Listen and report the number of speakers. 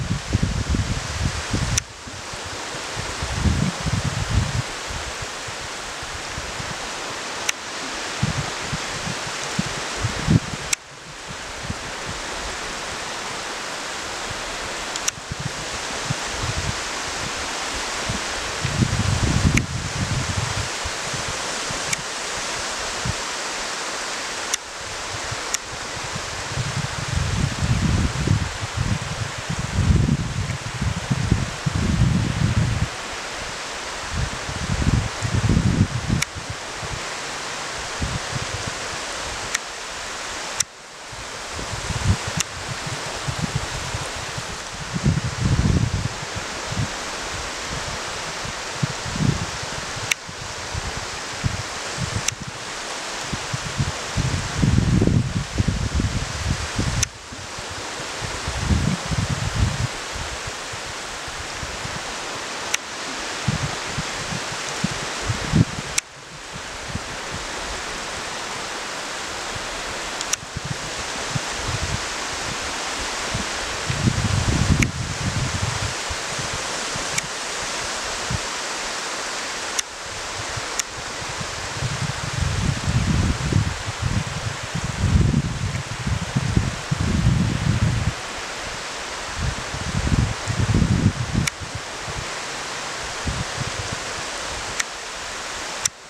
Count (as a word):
zero